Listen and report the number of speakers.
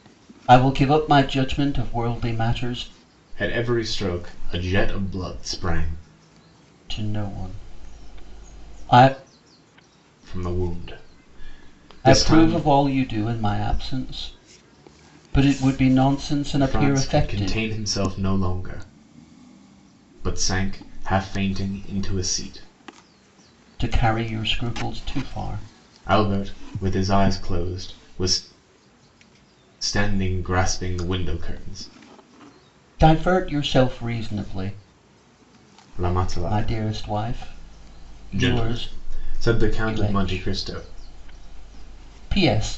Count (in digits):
2